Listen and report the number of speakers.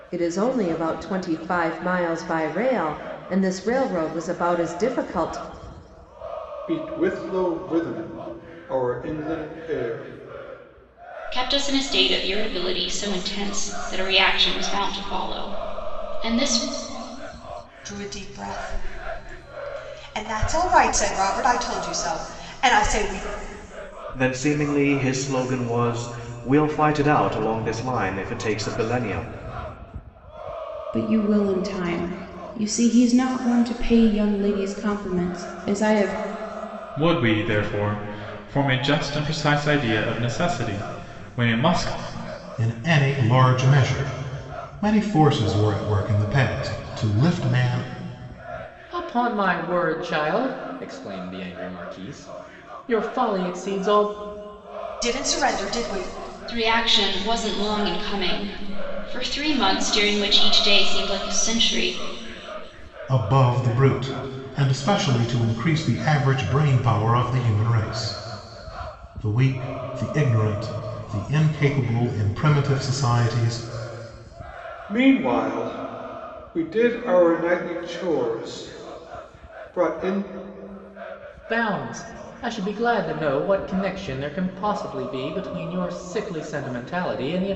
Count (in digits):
9